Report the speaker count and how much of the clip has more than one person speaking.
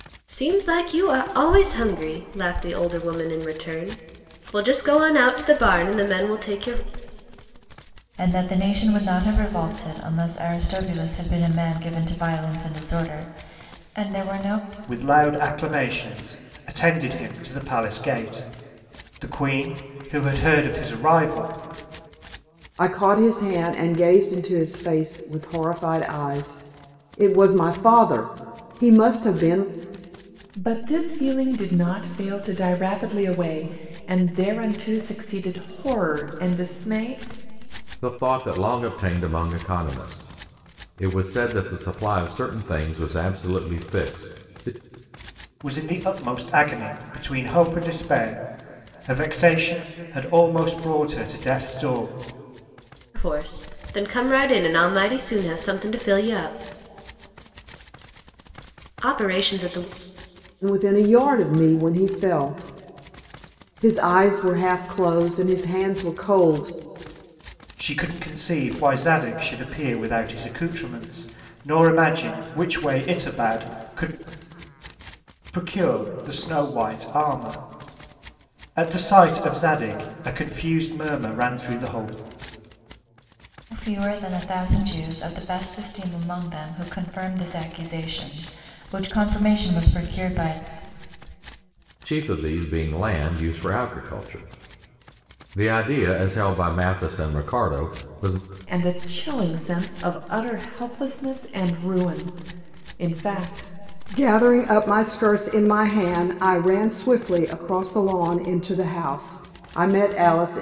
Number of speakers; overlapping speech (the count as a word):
six, no overlap